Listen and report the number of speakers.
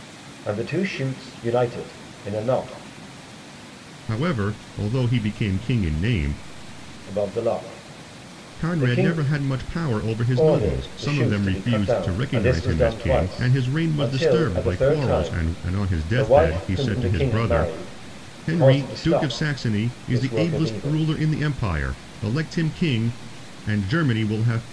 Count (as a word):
two